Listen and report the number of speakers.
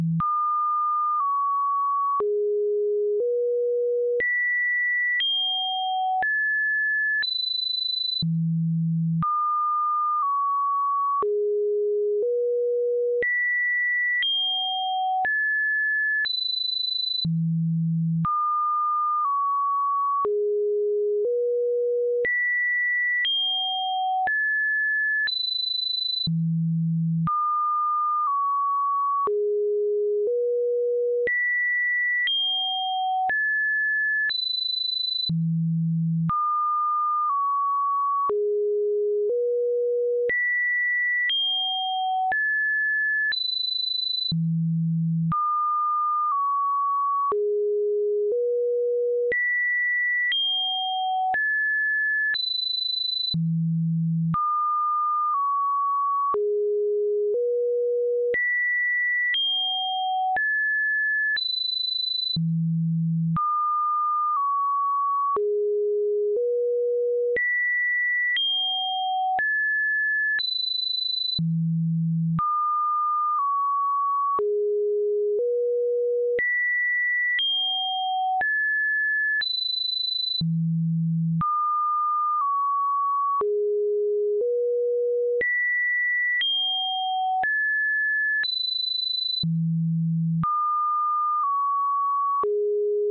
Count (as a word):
zero